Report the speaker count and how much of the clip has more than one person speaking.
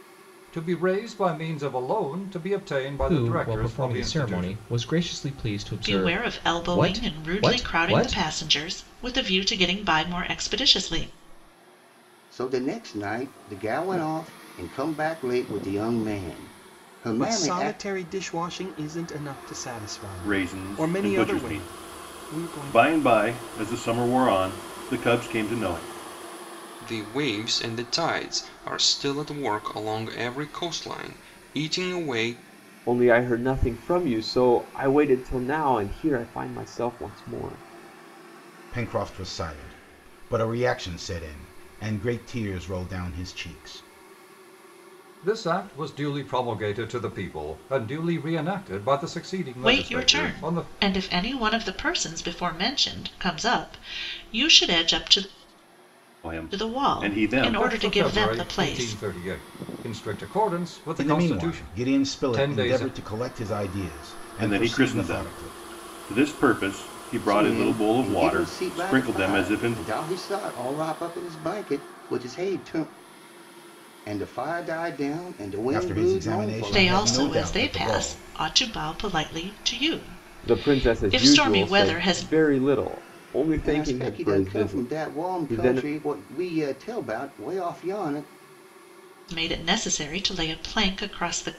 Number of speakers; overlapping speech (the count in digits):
9, about 26%